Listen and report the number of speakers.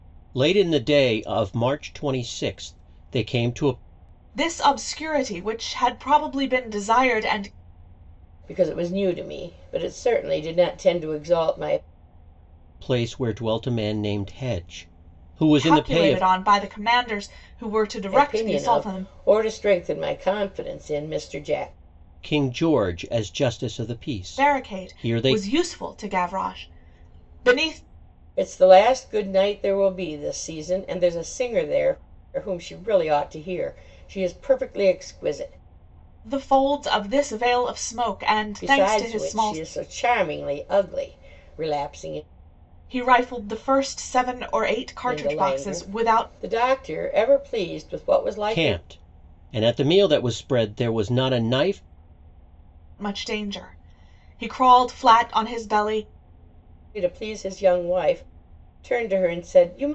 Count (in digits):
3